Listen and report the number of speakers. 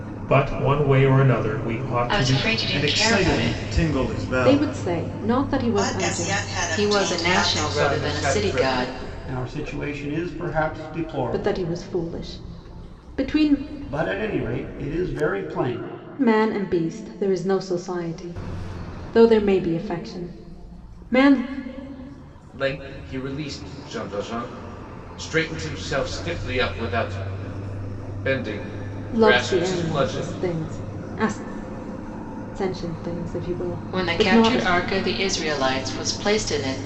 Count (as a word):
eight